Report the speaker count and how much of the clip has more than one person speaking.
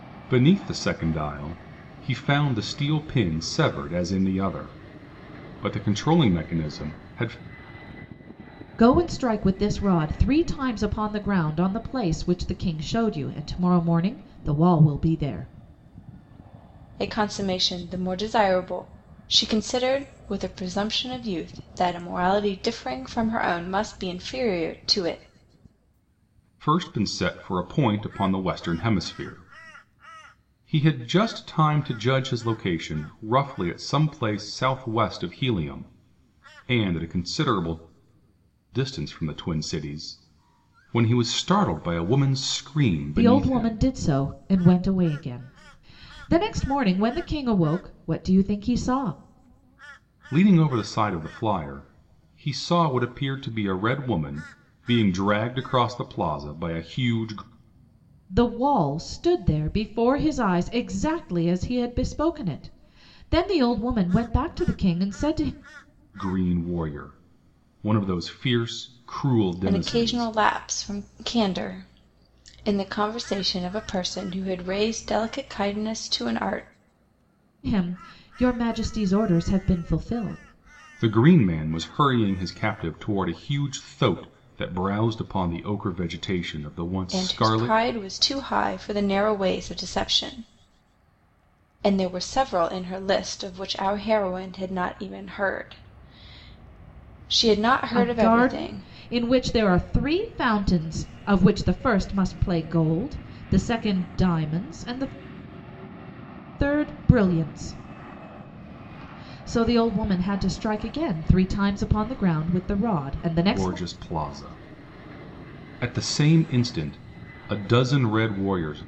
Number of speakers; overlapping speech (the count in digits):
3, about 3%